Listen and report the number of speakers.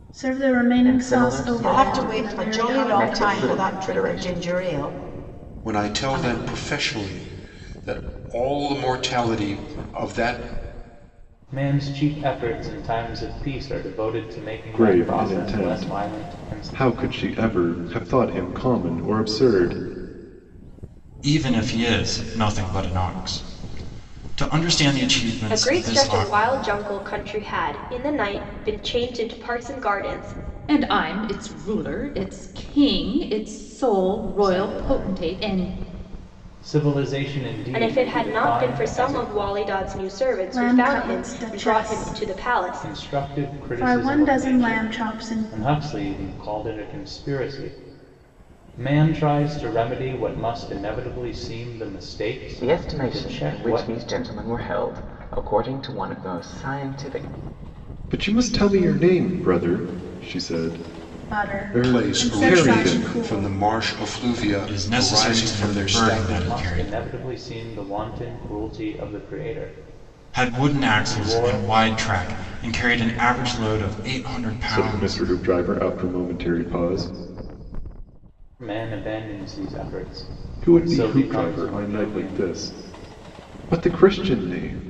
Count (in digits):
9